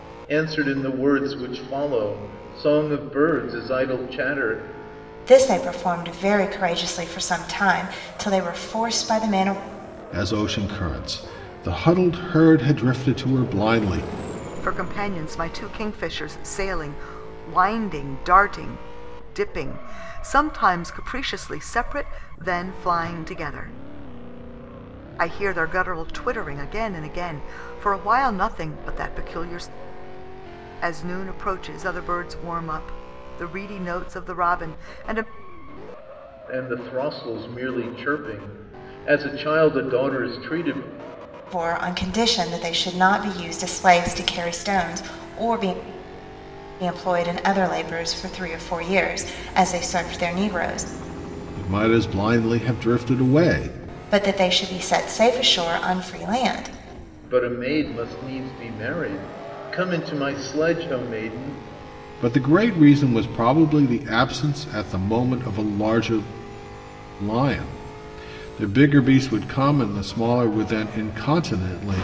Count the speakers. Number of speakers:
4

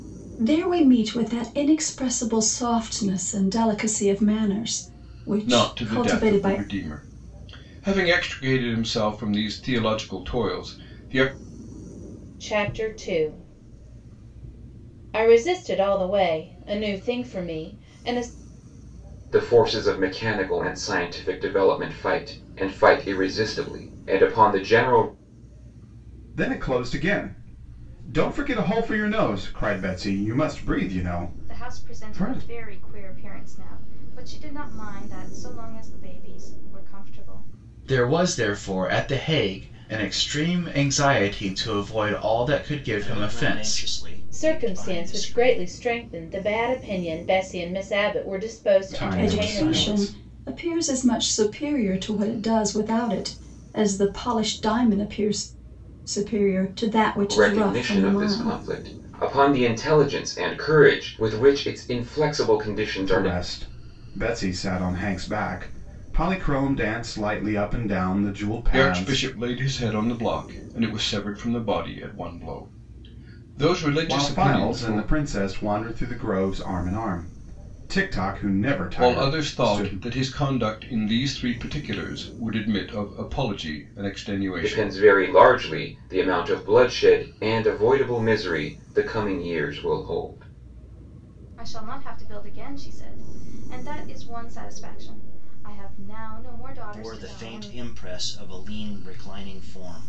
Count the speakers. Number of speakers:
8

